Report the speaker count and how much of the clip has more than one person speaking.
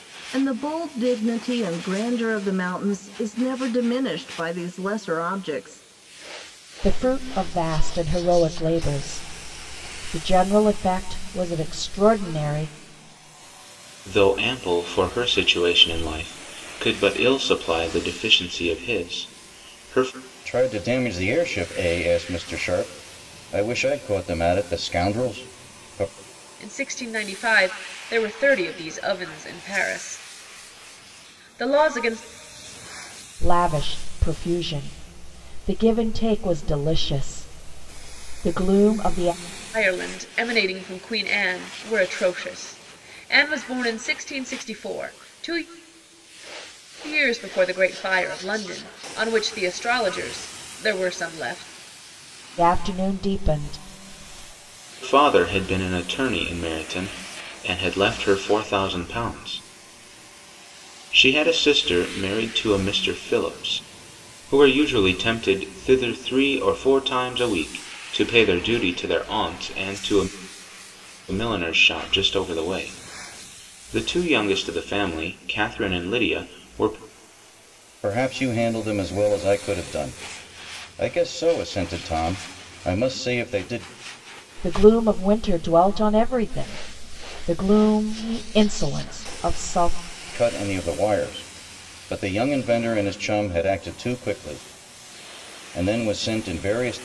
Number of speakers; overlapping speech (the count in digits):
5, no overlap